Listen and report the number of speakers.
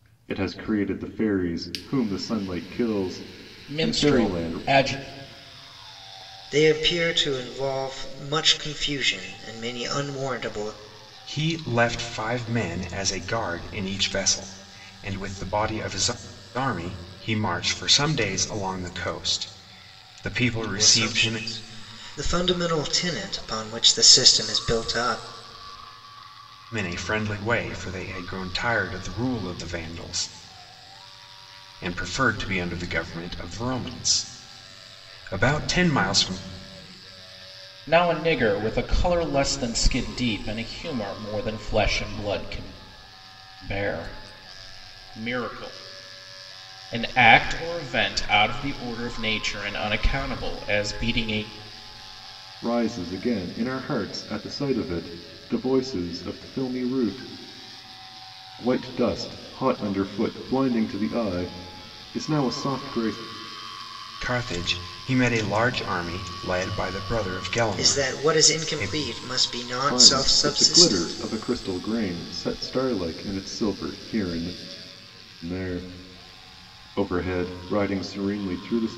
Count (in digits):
4